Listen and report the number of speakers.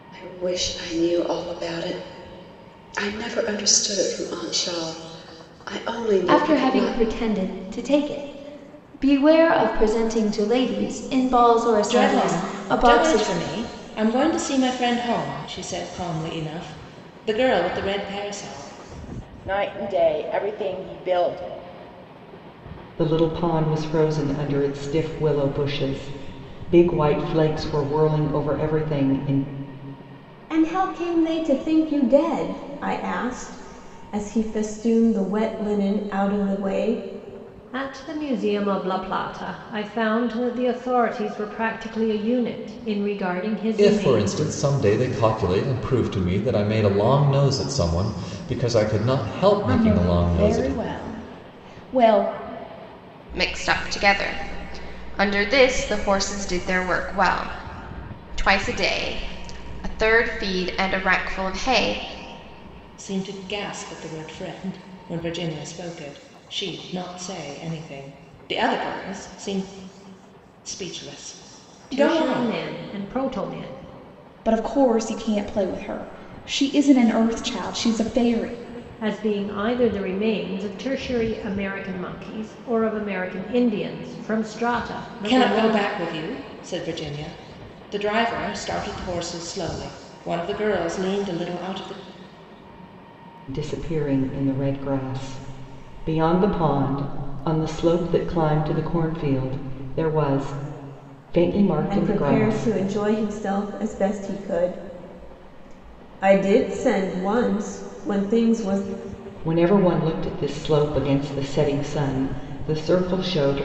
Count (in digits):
10